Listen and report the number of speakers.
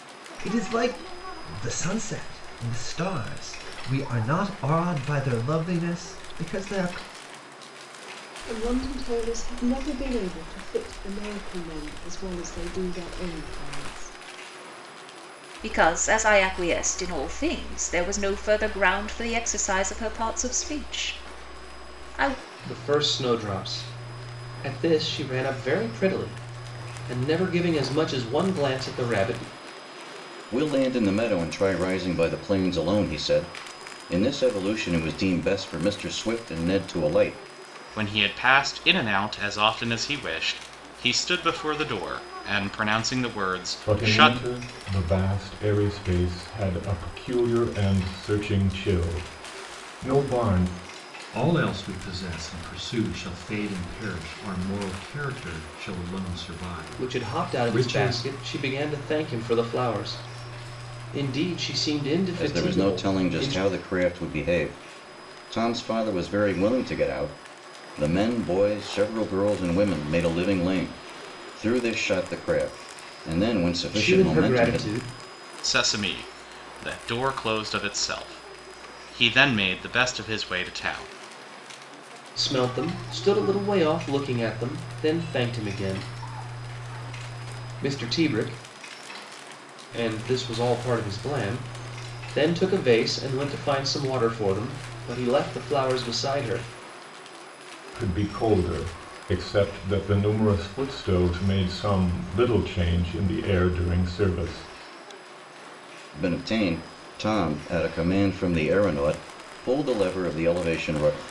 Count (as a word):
eight